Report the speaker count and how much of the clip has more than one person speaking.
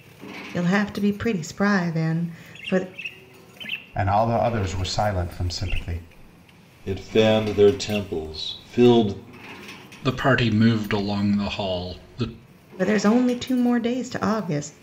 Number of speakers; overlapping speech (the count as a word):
four, no overlap